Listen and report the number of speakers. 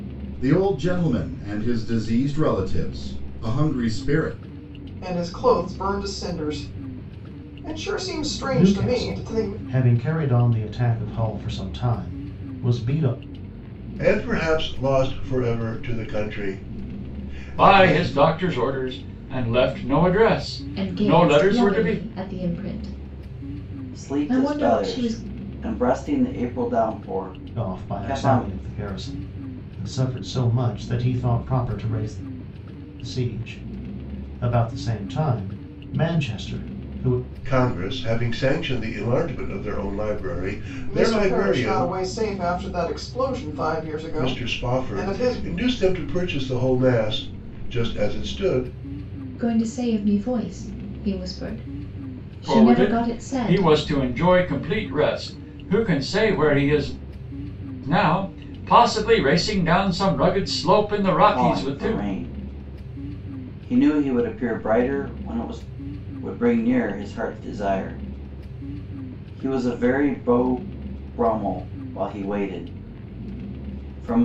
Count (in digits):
7